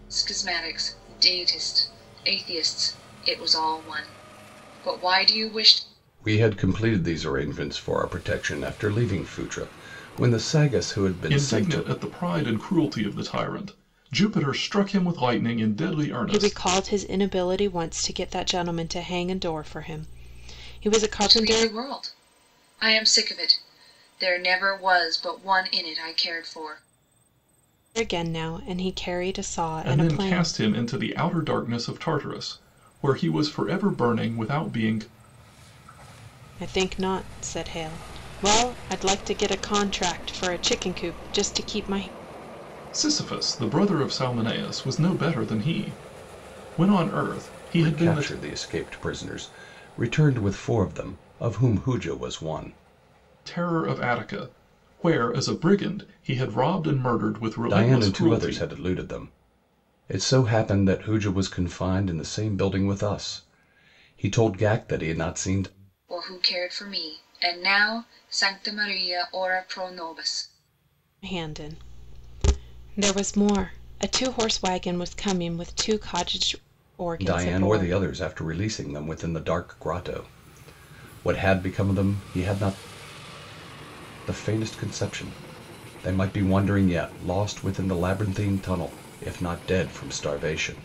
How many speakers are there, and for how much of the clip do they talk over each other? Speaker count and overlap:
four, about 5%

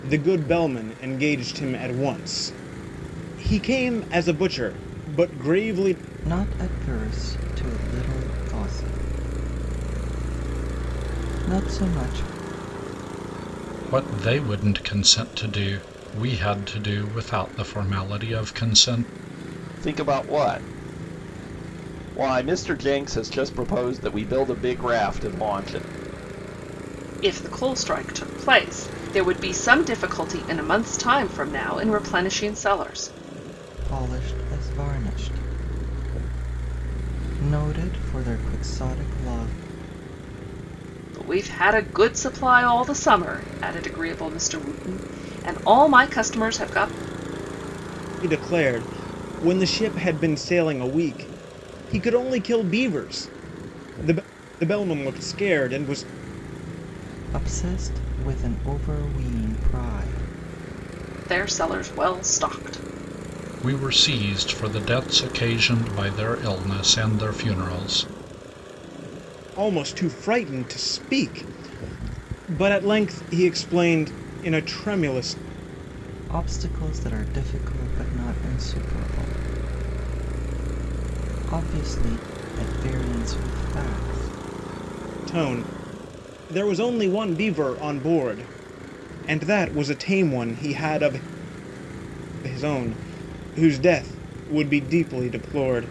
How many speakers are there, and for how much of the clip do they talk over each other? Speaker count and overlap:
five, no overlap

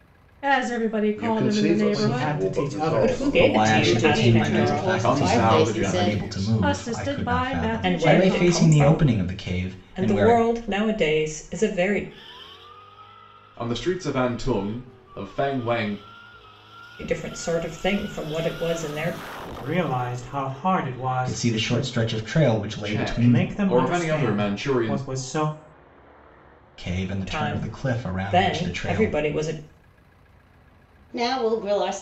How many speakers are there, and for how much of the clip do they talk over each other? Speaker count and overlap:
seven, about 41%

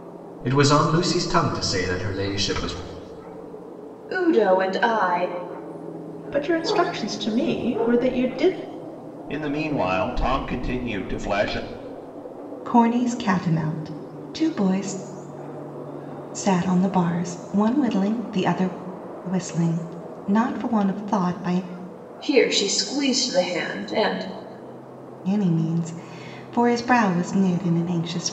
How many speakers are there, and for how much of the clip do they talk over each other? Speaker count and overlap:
five, no overlap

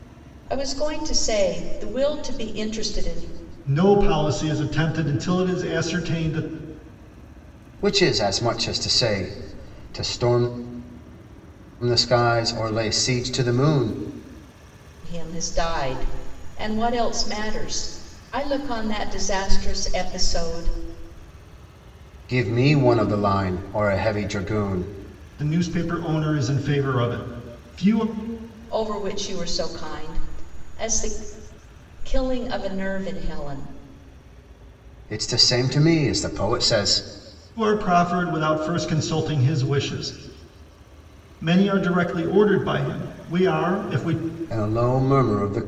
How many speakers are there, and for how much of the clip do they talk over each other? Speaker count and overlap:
three, no overlap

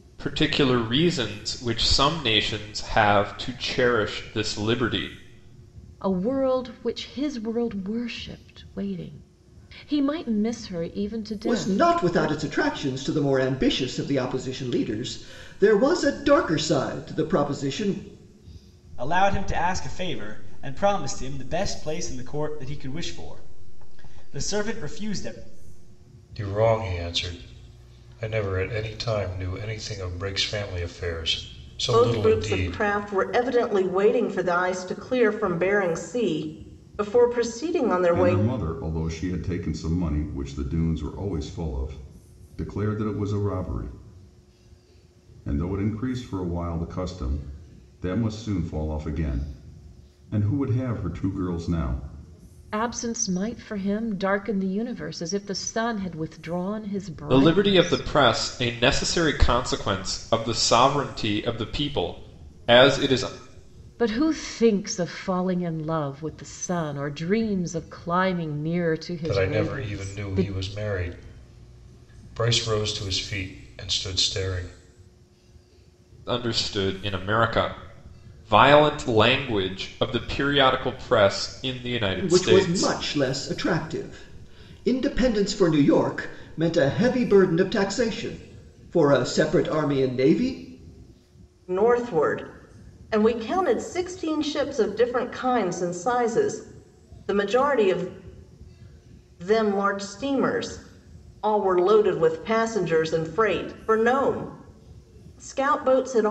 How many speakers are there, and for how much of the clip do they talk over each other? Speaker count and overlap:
seven, about 5%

